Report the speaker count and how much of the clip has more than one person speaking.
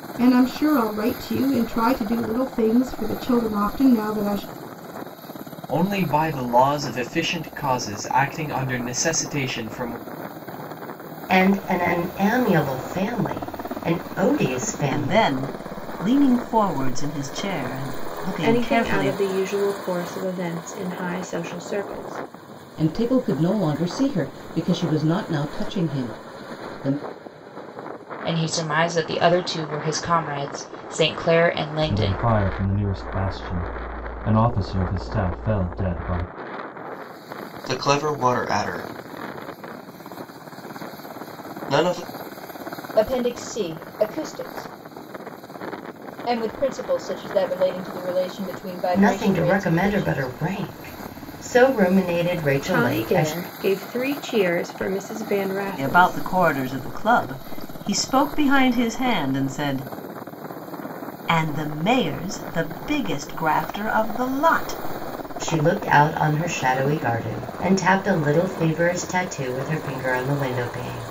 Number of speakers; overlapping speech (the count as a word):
ten, about 6%